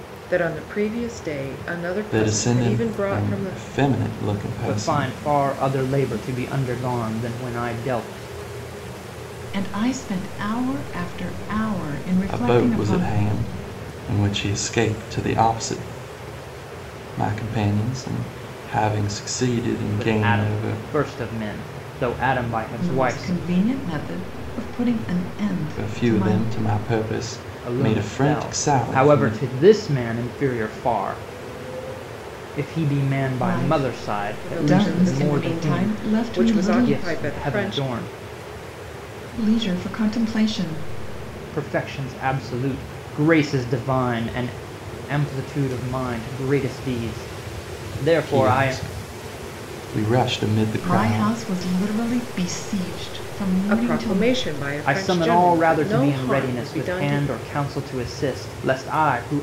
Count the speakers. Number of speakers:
four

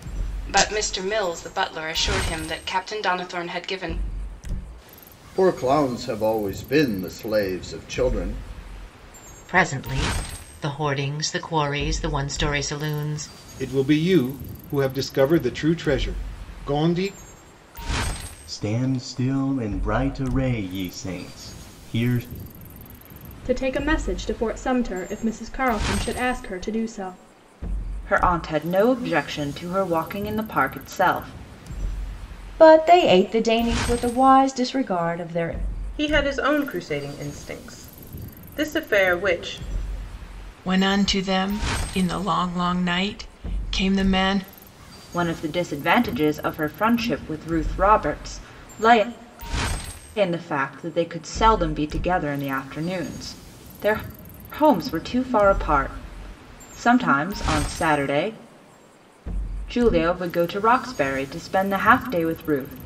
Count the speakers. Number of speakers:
ten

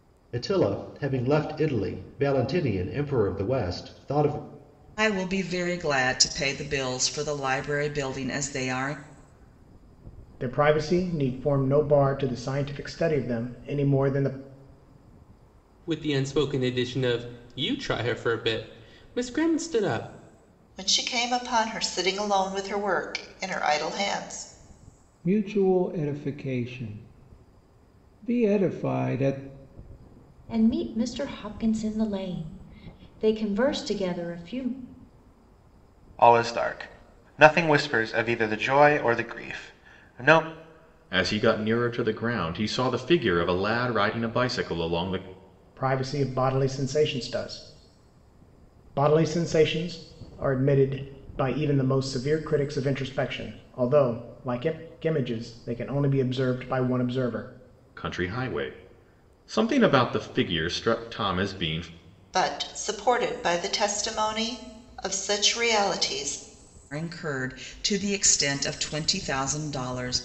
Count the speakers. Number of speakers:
nine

